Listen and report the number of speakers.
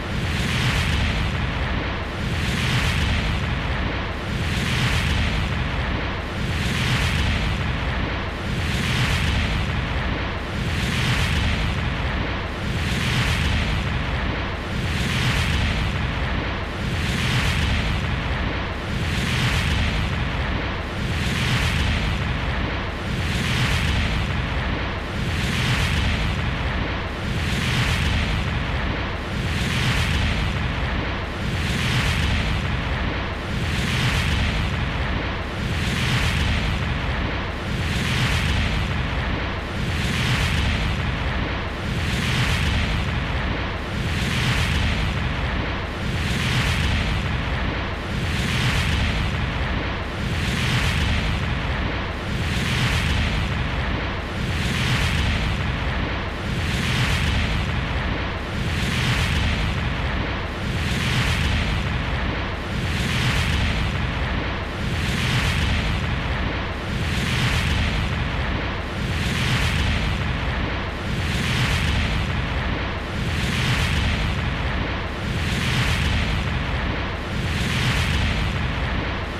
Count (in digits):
0